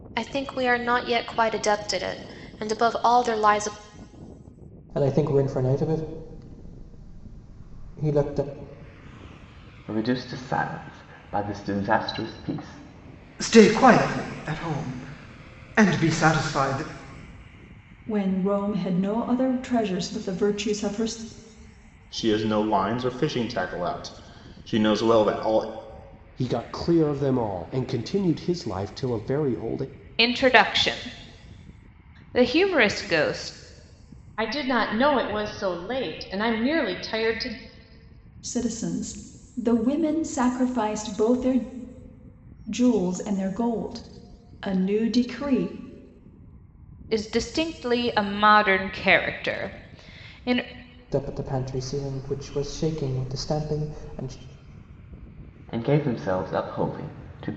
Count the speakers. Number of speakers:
9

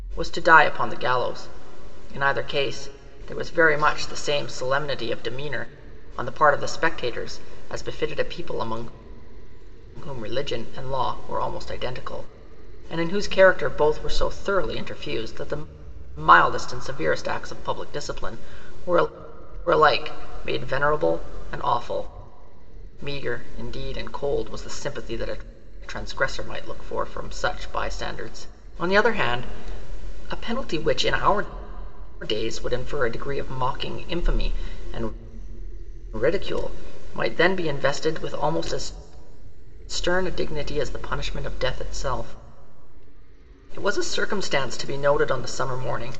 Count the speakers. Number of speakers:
1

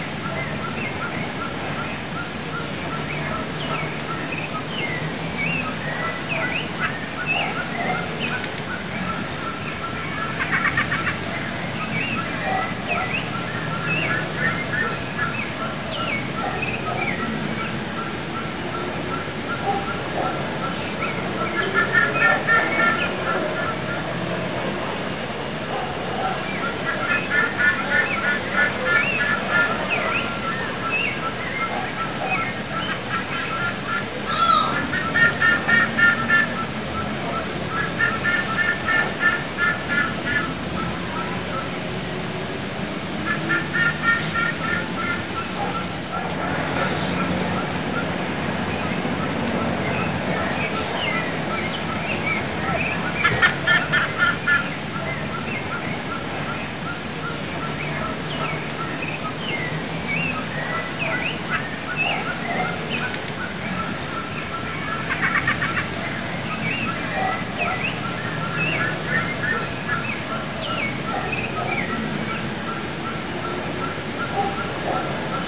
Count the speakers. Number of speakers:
0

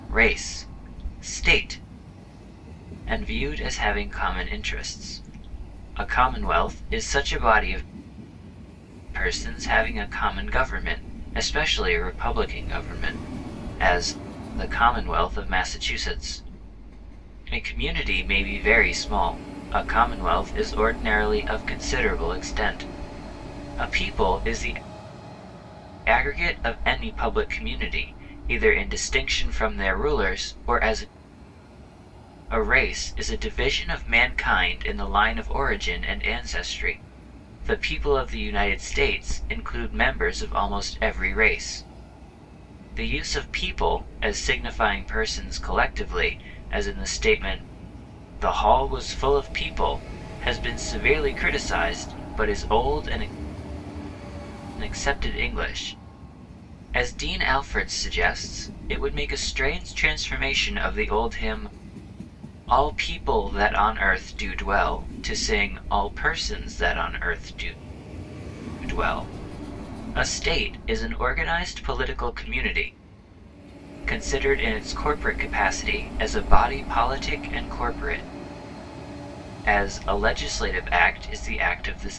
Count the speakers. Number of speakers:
1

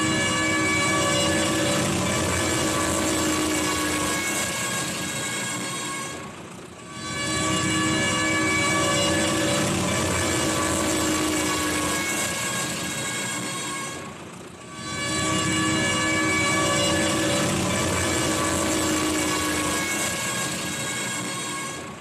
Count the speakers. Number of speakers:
0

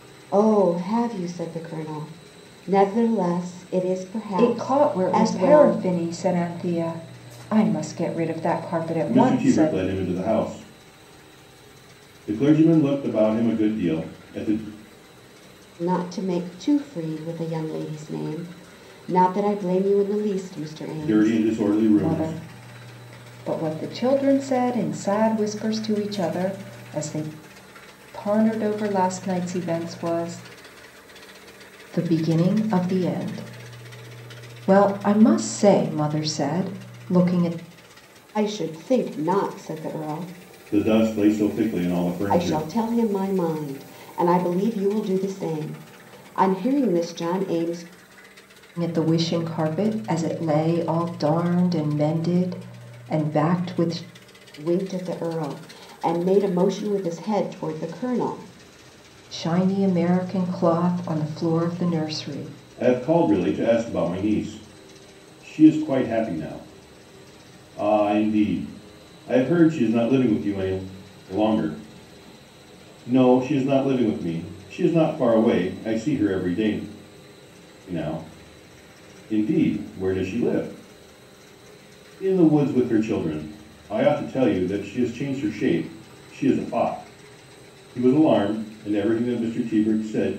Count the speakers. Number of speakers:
3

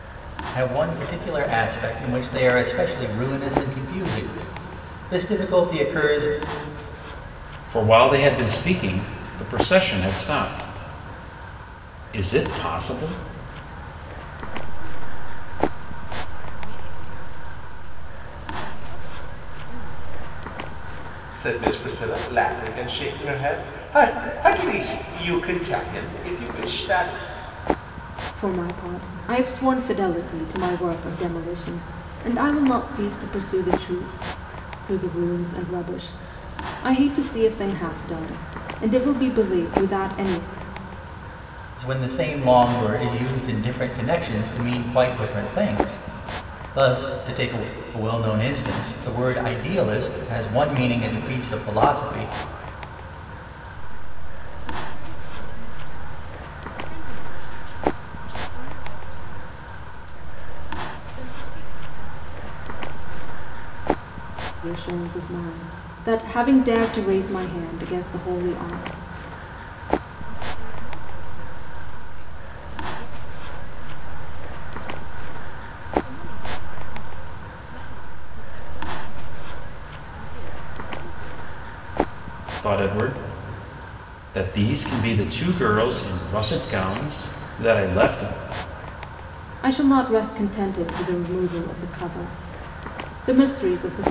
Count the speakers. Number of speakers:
5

